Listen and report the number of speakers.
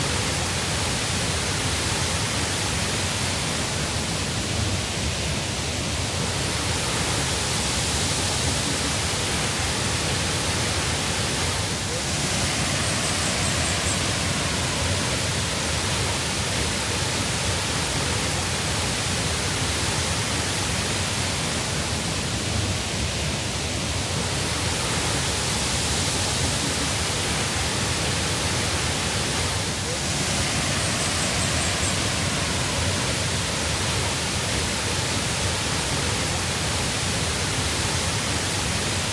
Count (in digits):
0